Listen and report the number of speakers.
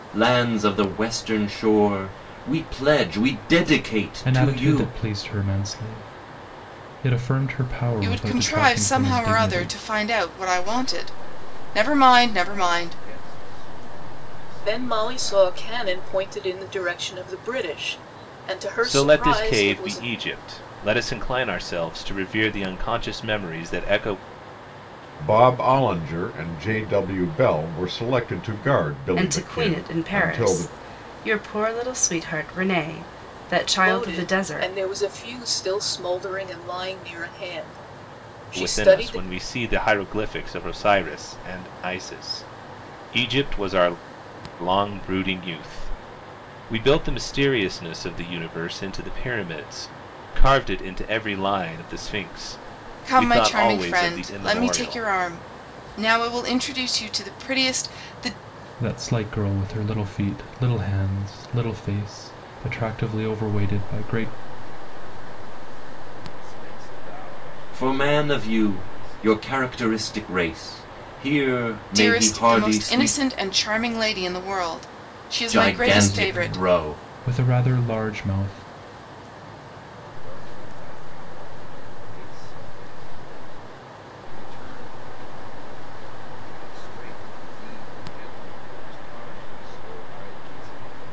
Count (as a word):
eight